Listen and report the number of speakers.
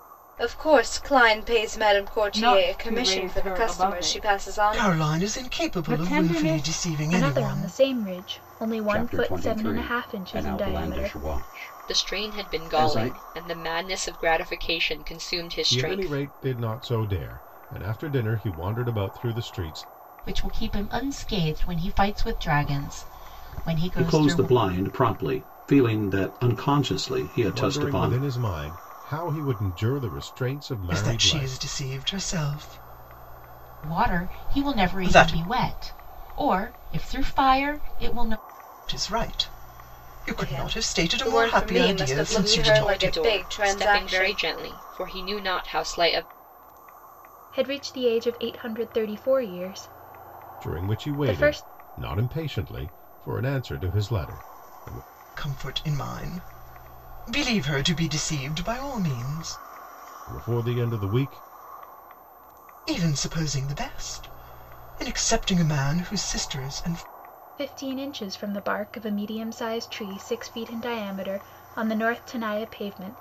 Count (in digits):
9